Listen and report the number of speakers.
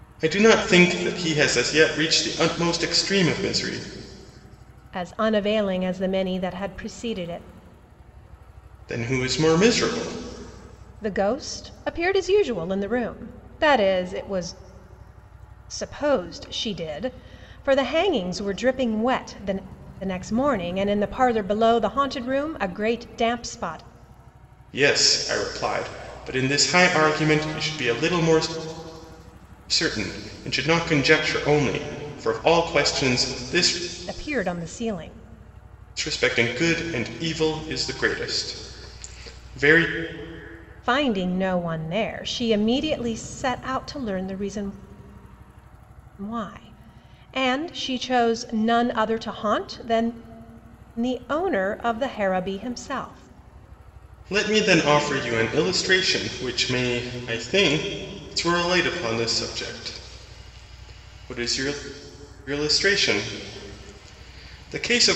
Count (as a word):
two